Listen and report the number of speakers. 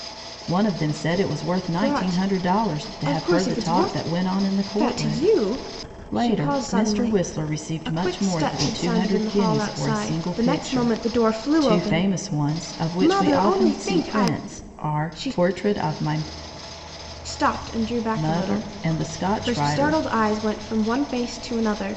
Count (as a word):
two